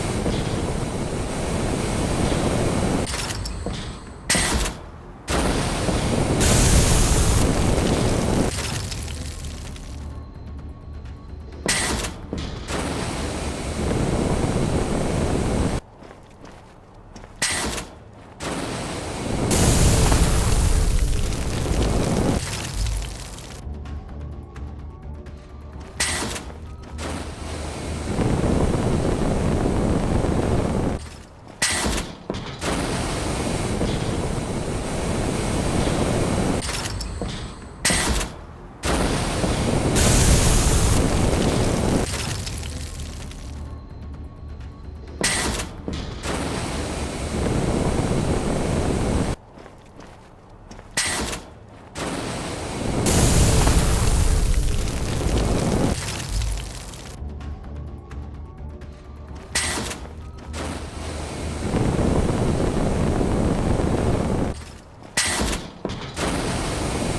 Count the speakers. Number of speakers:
zero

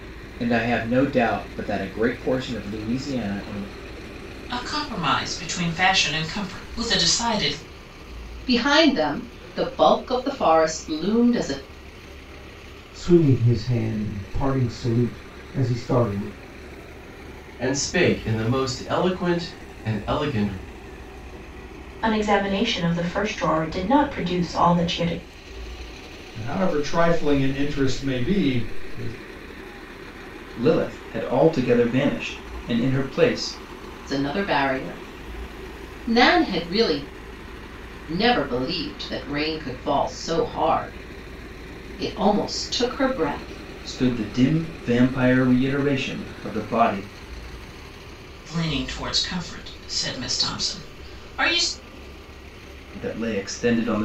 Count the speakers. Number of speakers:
eight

